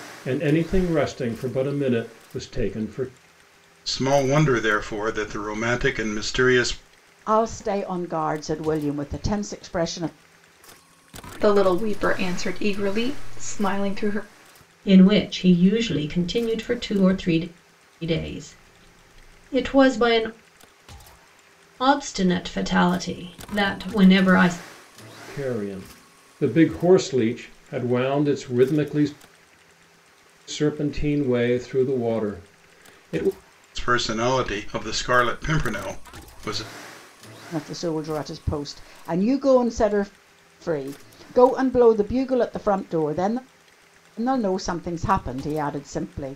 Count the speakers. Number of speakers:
five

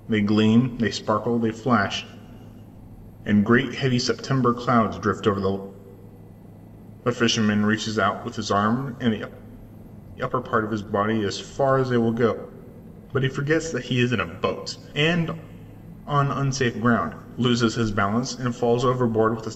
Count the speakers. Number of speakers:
one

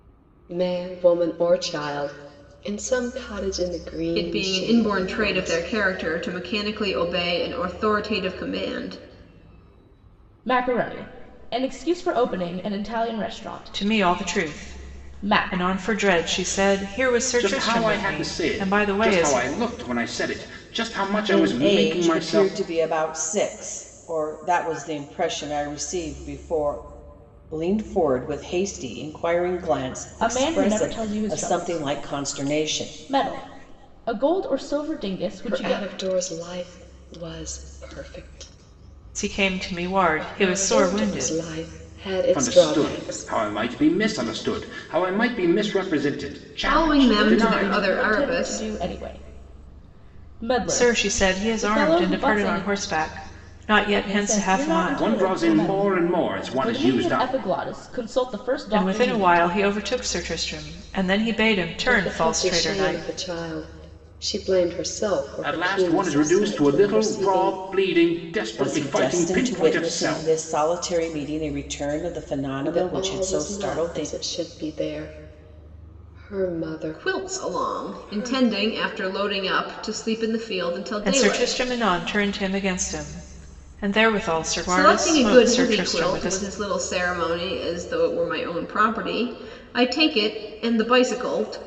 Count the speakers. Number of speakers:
six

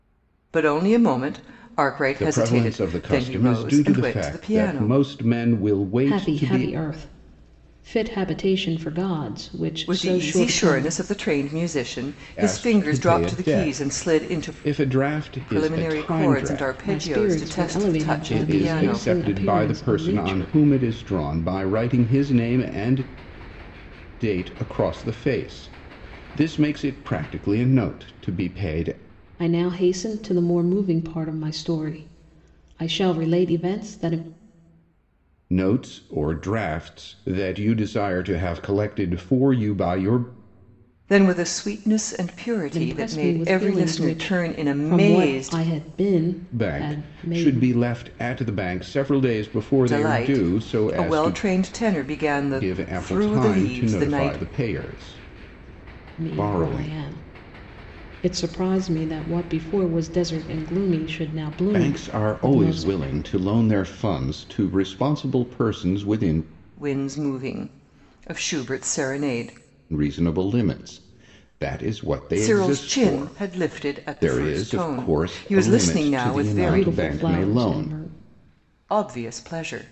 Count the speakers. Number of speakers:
three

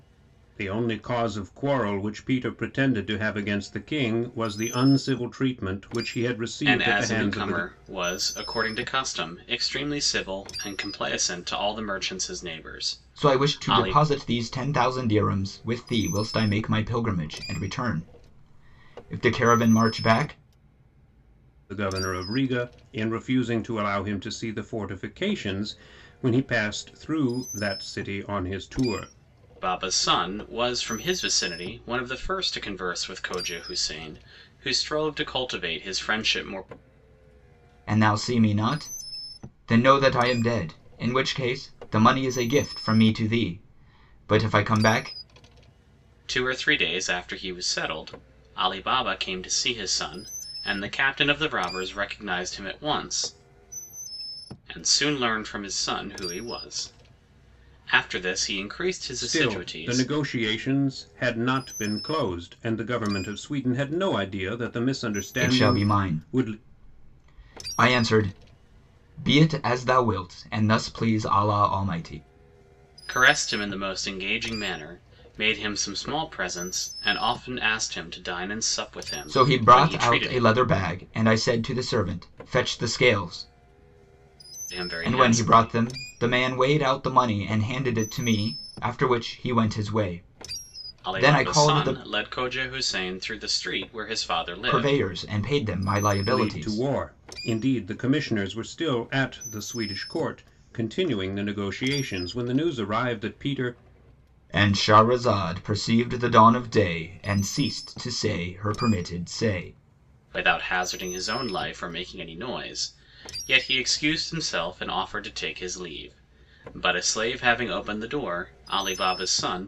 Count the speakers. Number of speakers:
three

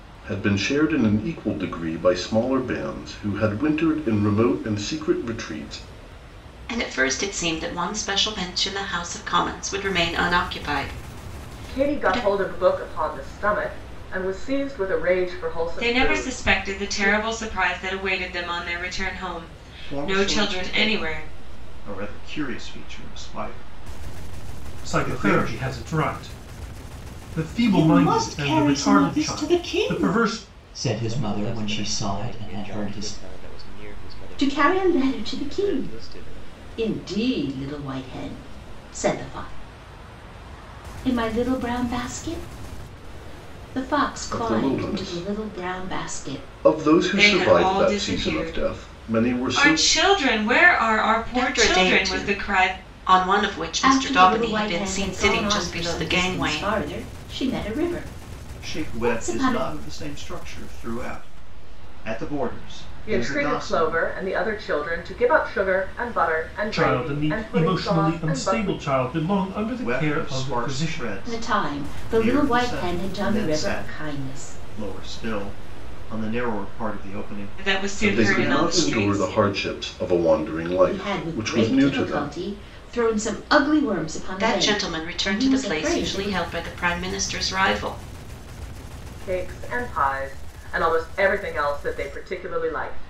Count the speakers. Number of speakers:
nine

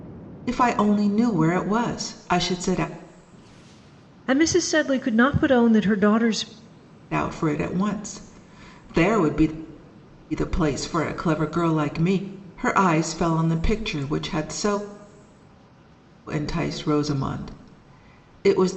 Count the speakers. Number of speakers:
two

